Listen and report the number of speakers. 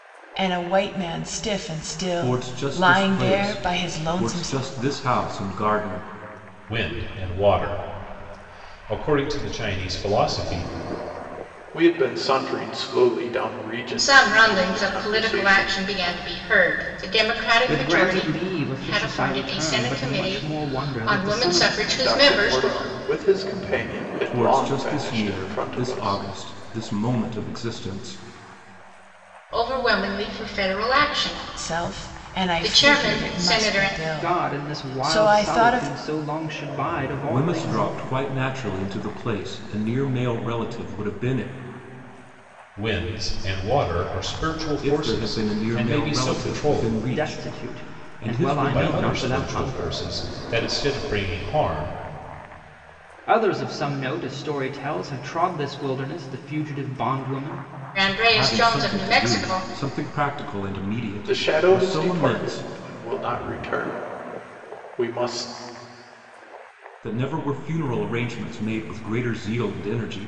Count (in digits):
6